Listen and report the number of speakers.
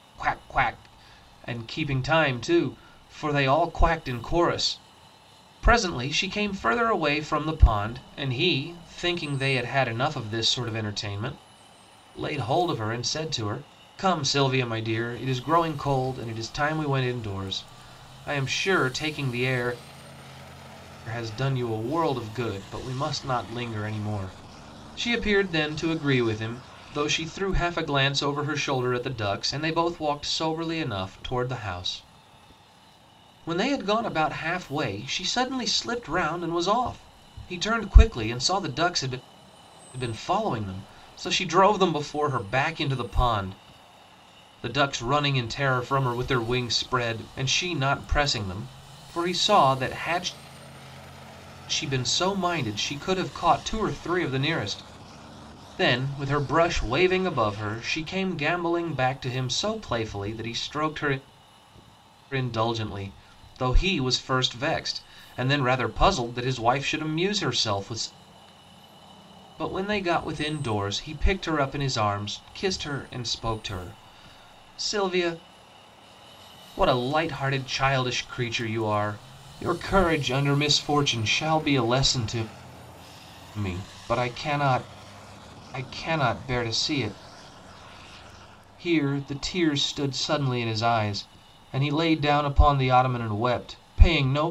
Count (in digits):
1